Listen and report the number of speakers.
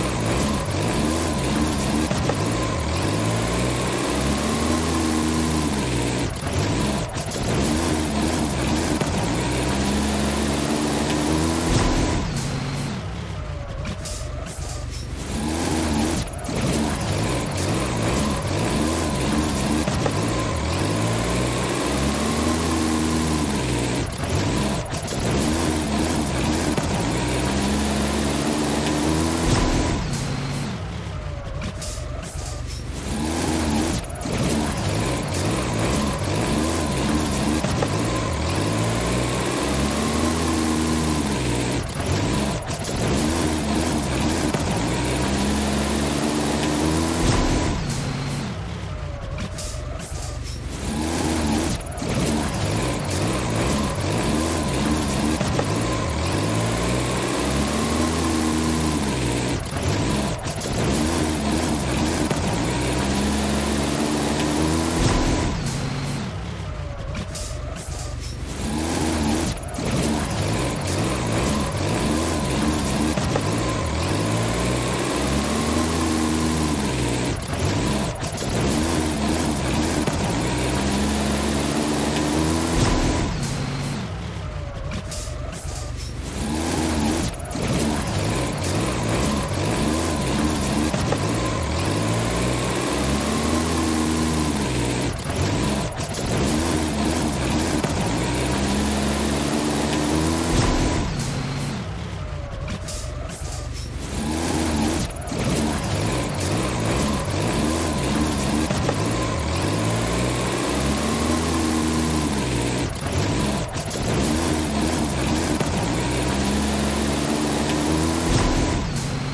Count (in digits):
0